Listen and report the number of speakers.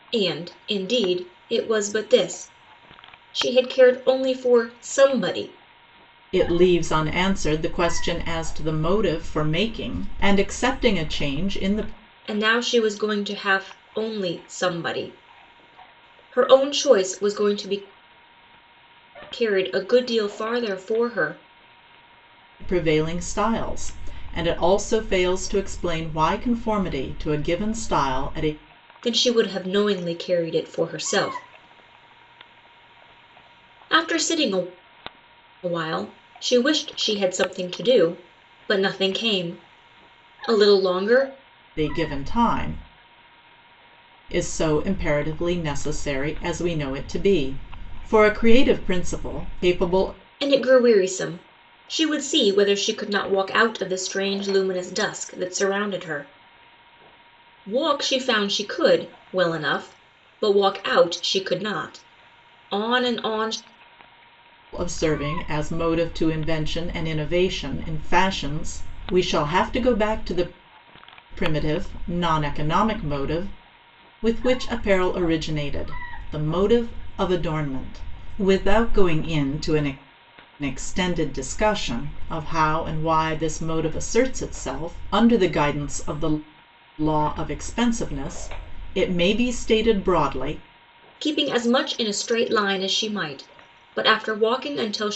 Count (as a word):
two